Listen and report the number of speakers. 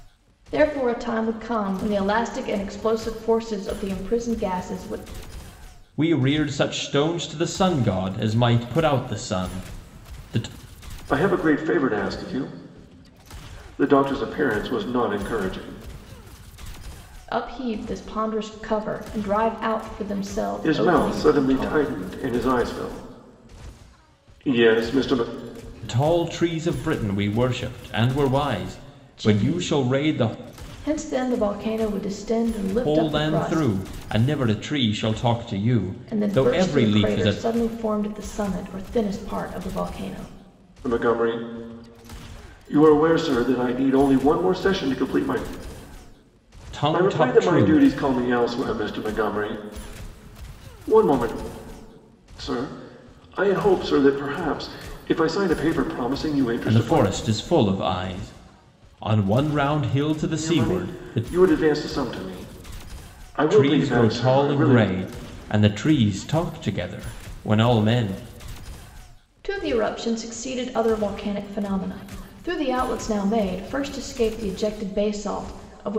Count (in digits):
3